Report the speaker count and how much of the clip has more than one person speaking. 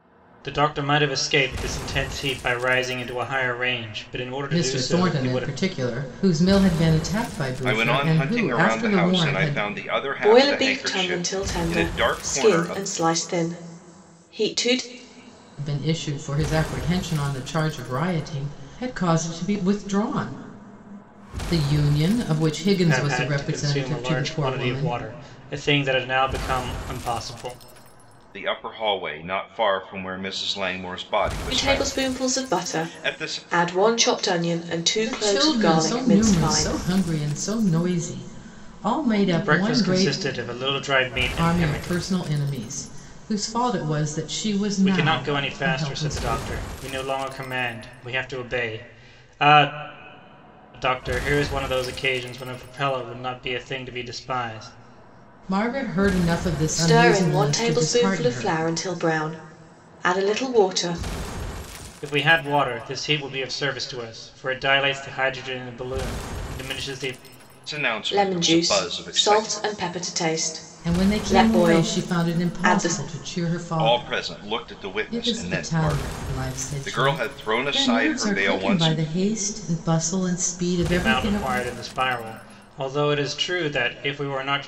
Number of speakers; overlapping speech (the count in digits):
4, about 31%